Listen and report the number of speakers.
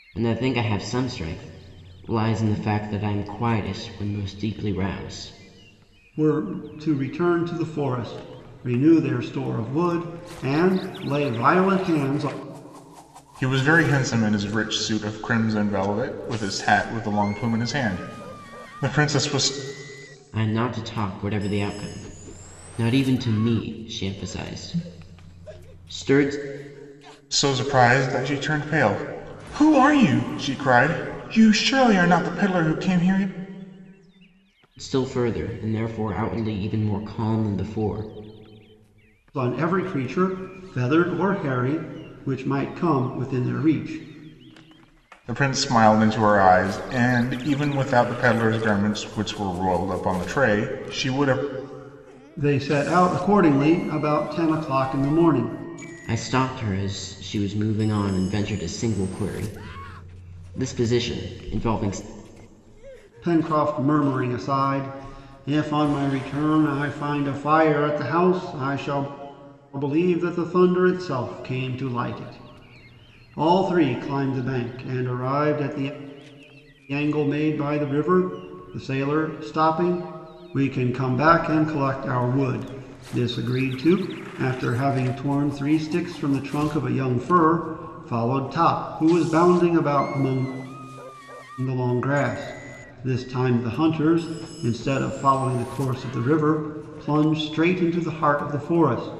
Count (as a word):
three